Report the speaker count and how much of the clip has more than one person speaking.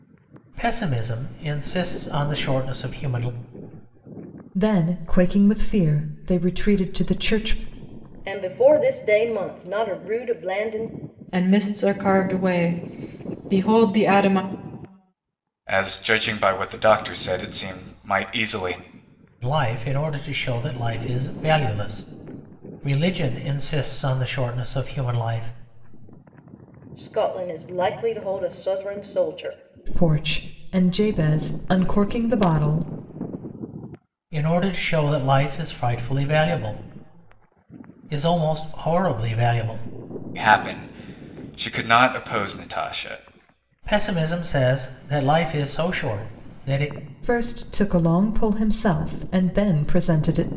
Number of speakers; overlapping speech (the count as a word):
five, no overlap